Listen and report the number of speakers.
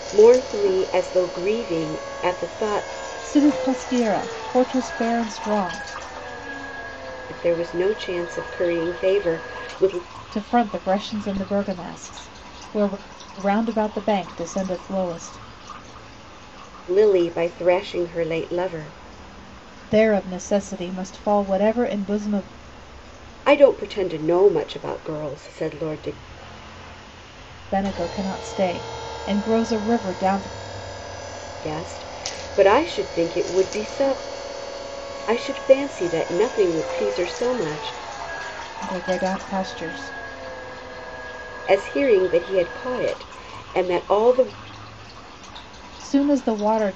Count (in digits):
2